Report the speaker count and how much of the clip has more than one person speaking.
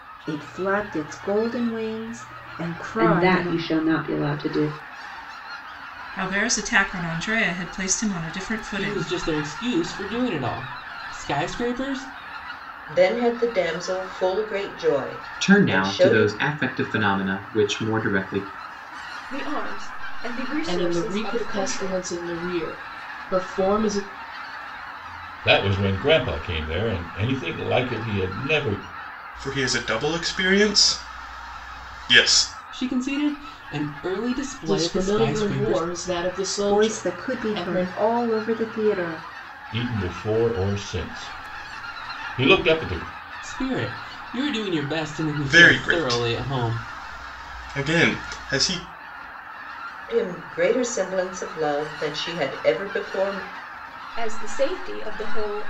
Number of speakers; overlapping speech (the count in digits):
10, about 13%